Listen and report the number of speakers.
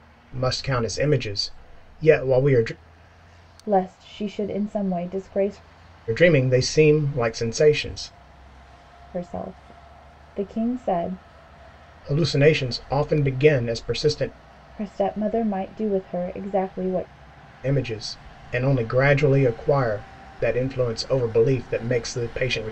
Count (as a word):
two